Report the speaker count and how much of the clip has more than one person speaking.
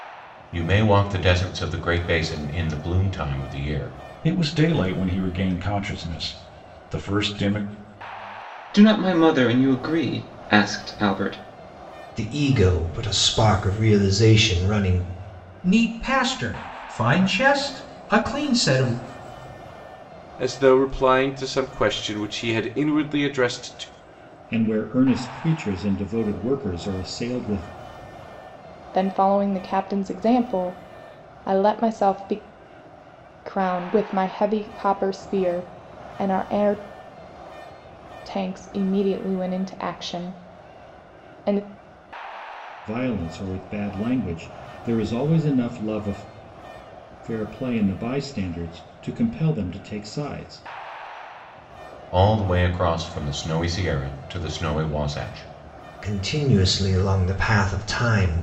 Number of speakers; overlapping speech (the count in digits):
8, no overlap